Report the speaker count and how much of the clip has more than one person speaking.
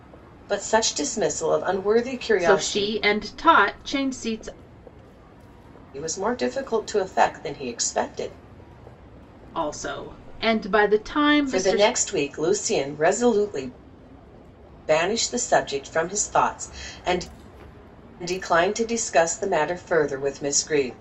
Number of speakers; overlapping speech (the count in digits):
2, about 5%